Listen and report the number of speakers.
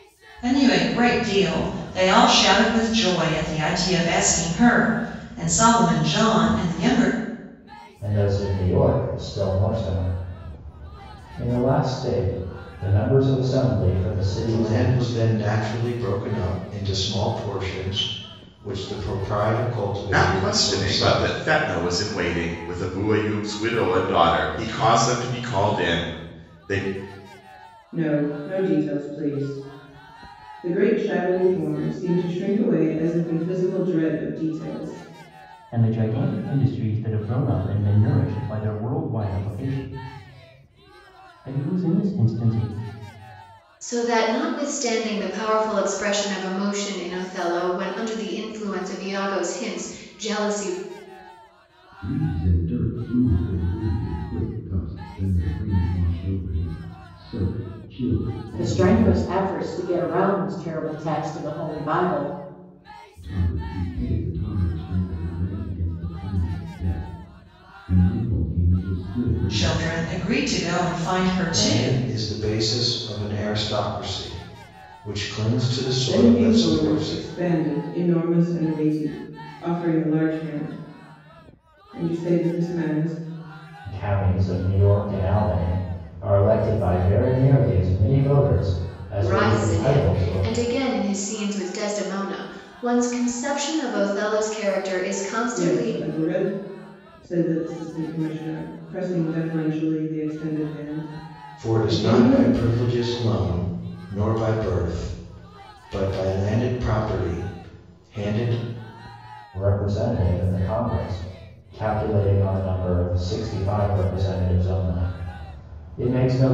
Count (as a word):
nine